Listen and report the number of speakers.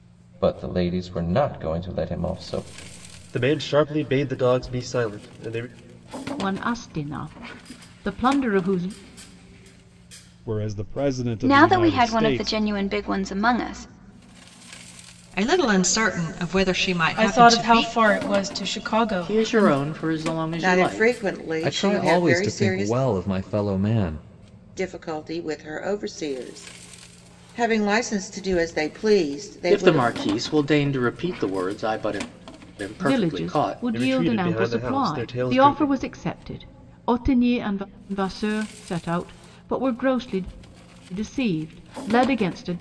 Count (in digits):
10